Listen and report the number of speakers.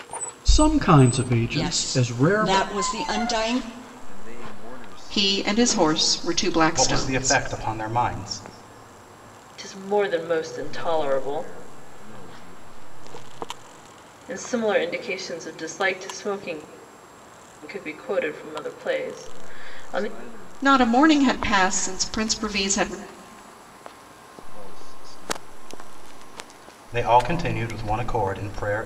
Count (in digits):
6